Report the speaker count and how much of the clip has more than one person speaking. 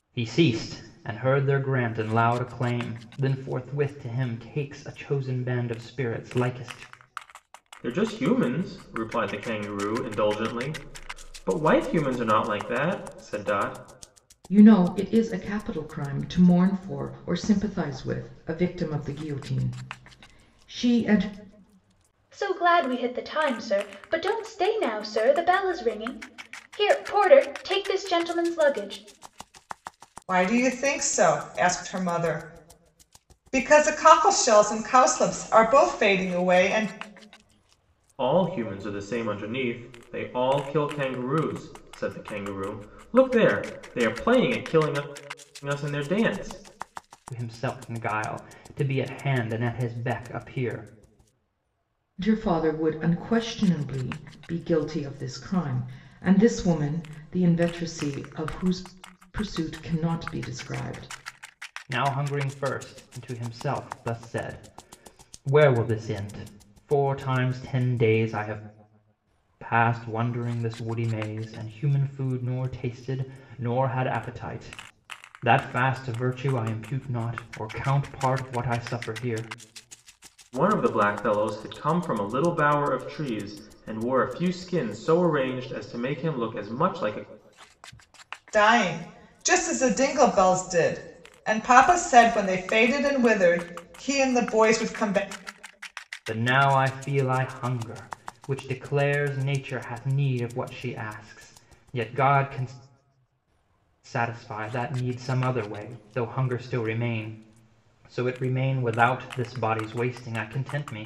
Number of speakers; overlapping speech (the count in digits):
5, no overlap